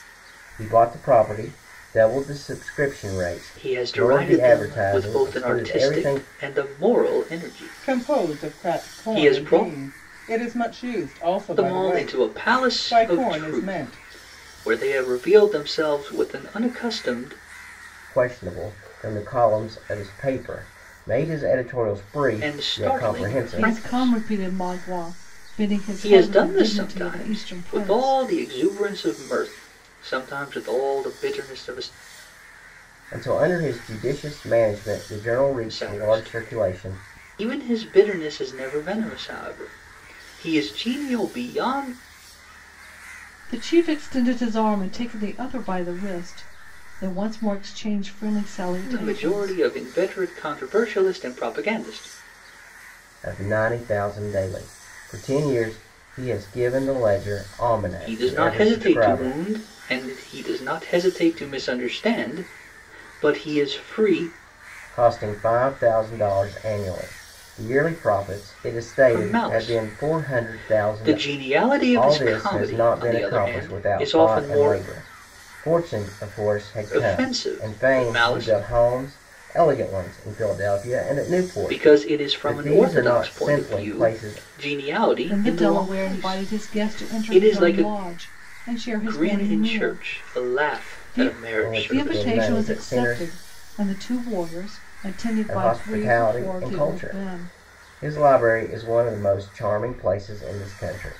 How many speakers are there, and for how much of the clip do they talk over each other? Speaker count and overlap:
3, about 33%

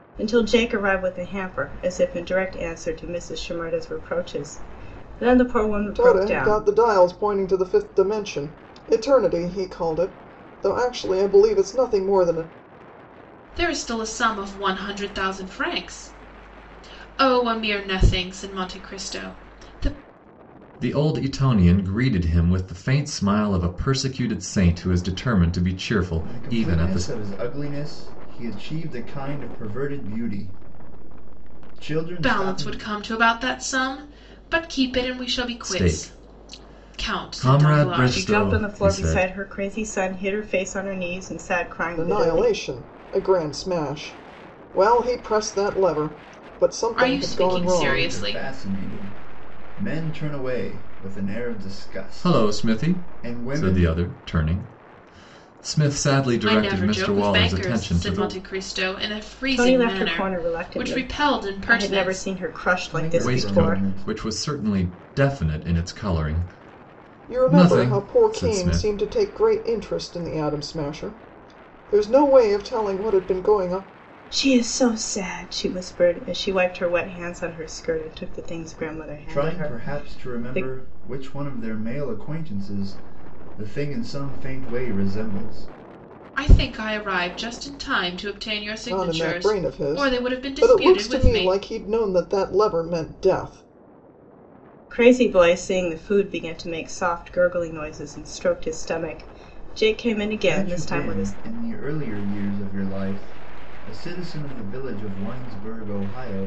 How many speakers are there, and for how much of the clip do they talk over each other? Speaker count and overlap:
5, about 21%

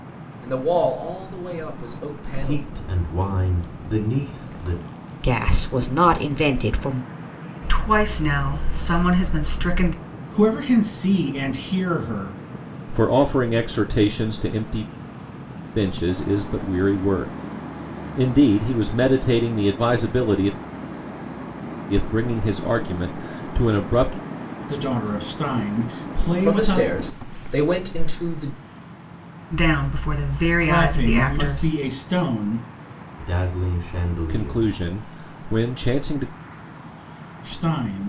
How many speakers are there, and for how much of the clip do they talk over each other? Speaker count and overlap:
6, about 7%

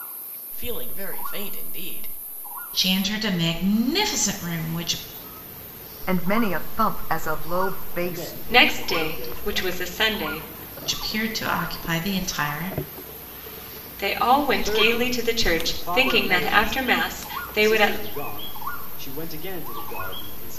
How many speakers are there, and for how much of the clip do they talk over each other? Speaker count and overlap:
5, about 22%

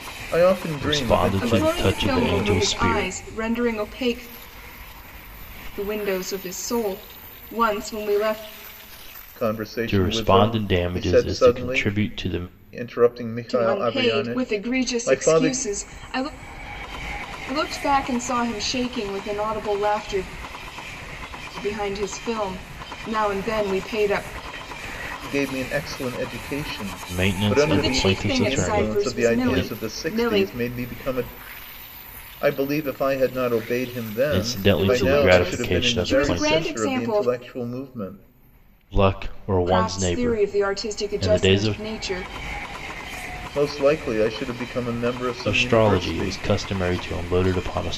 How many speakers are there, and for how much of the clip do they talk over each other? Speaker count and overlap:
3, about 34%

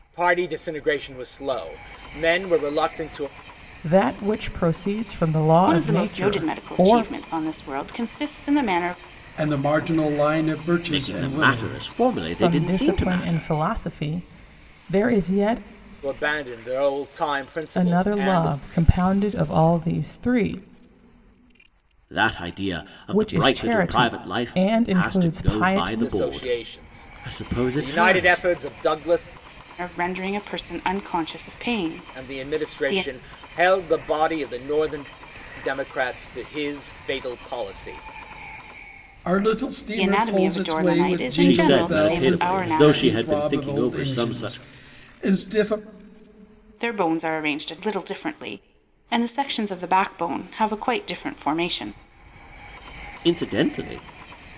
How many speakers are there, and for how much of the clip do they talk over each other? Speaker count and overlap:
5, about 29%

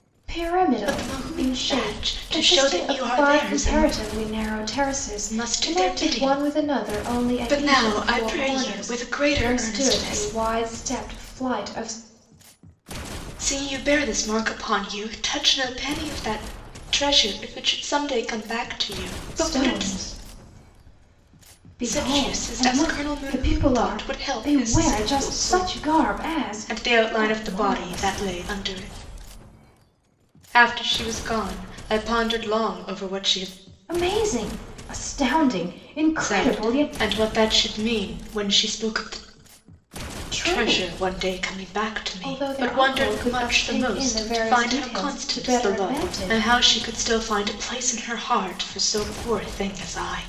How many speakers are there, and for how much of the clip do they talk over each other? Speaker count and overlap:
2, about 37%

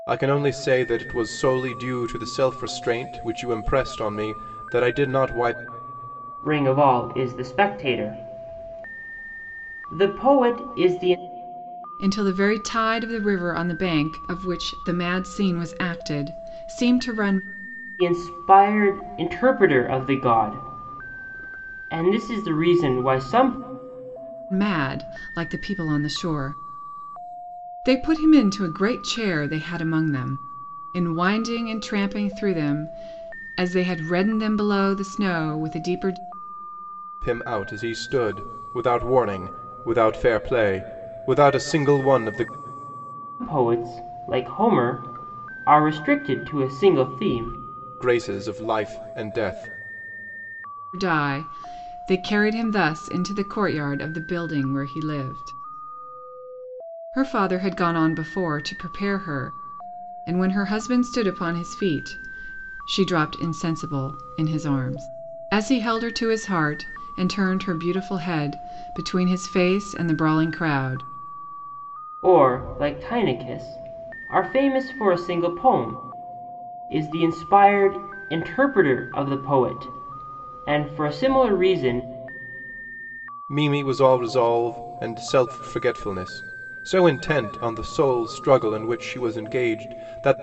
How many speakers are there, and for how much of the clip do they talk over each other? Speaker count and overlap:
3, no overlap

